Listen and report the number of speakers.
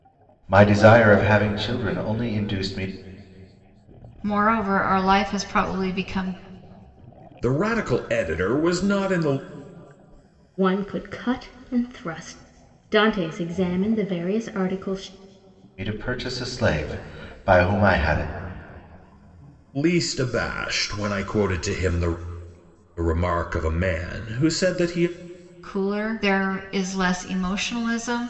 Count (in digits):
4